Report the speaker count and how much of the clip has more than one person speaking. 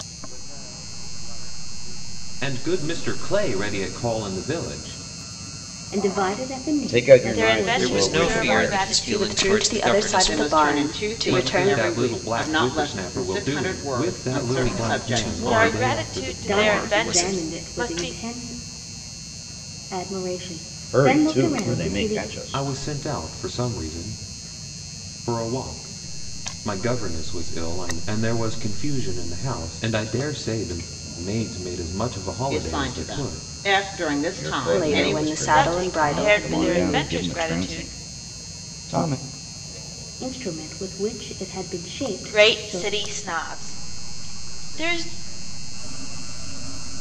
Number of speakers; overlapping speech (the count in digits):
8, about 51%